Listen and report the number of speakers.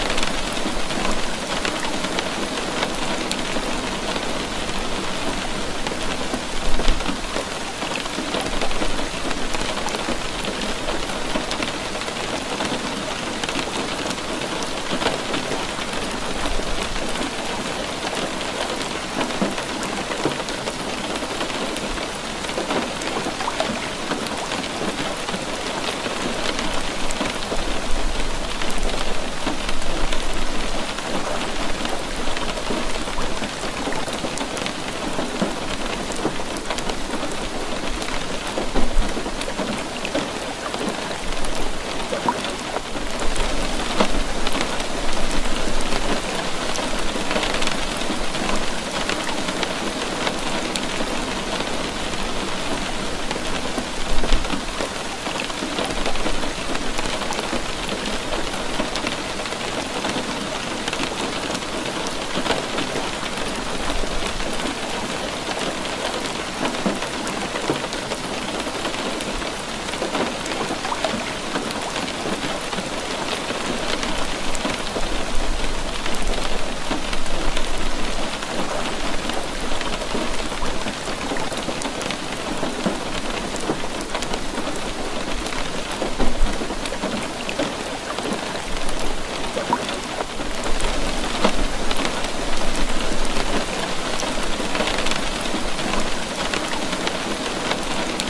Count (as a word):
zero